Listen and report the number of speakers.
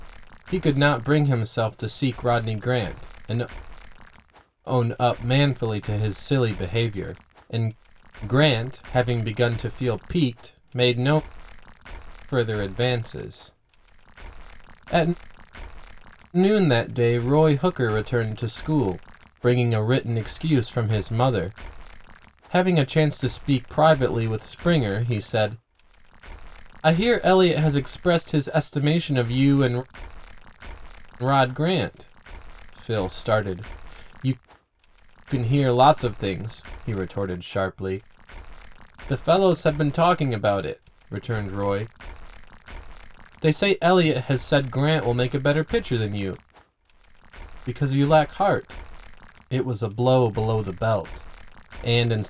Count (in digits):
1